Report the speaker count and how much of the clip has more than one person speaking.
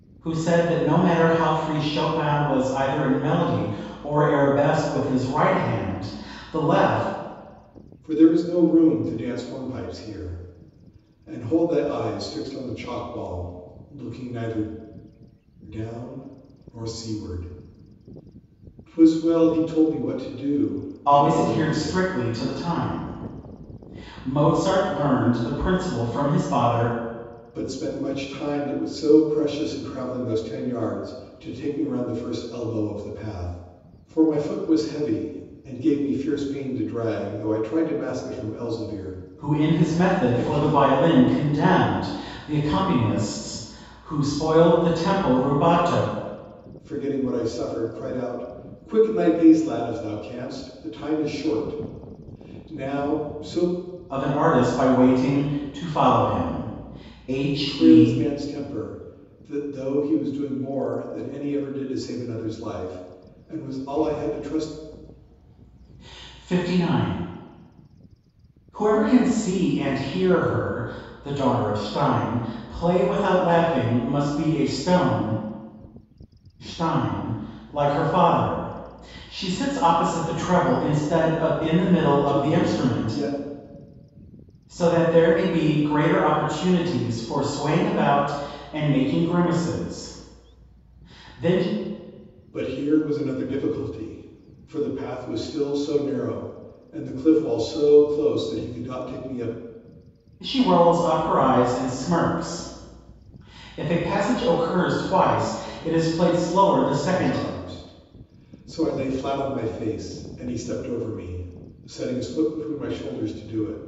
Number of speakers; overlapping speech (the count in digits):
2, about 5%